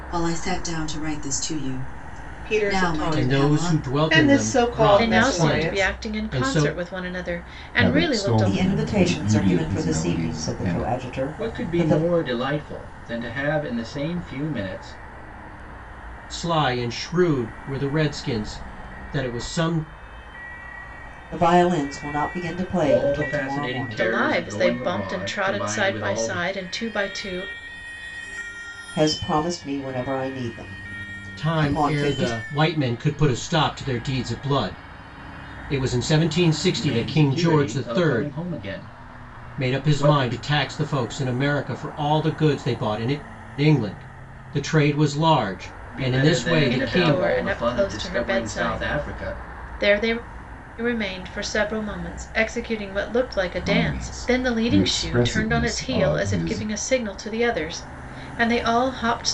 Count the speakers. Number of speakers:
7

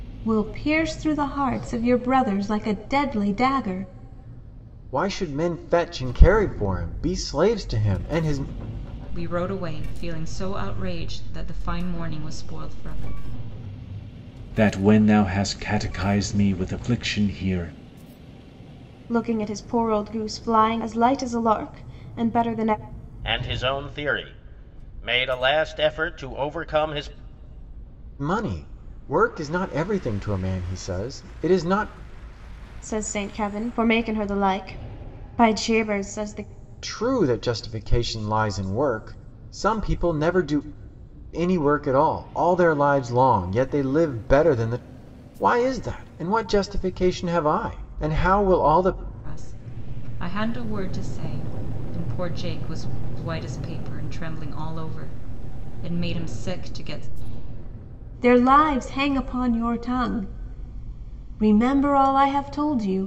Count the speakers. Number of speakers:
6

